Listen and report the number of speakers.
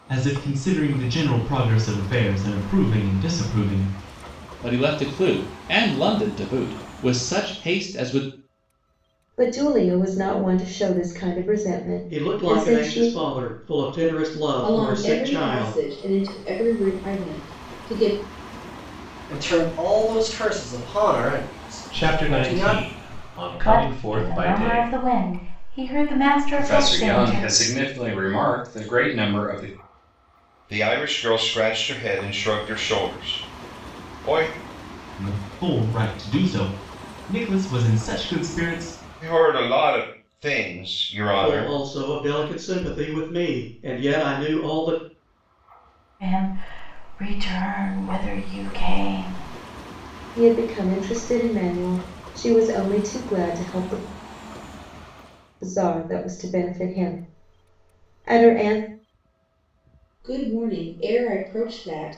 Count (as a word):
ten